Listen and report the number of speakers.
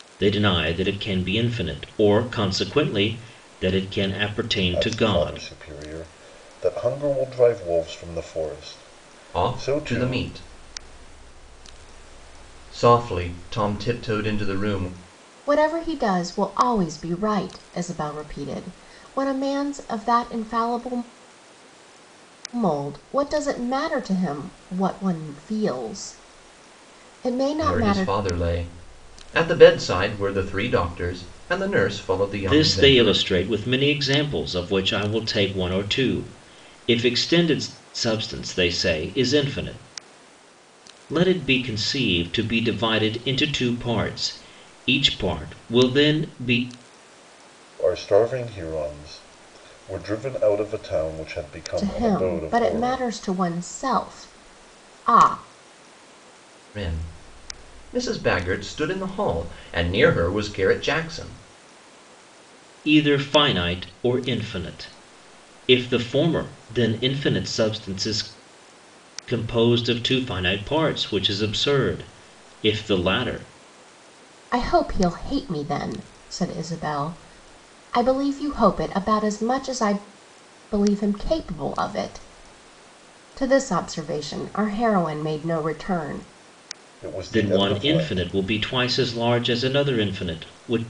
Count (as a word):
four